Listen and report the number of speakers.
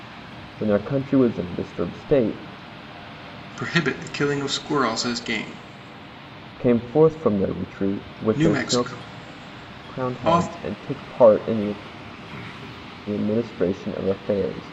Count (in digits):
2